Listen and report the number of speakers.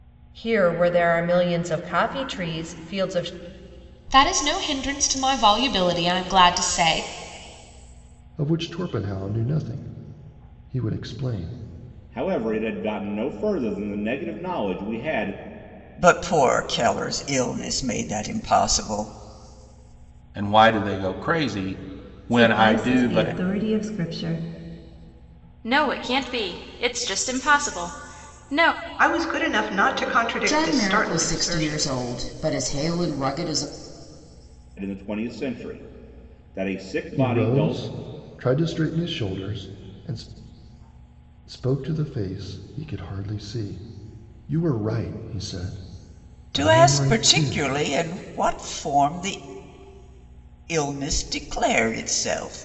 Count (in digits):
10